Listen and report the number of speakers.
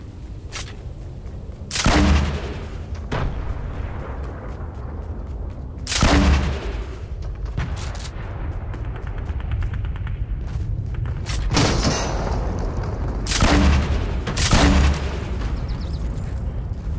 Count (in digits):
0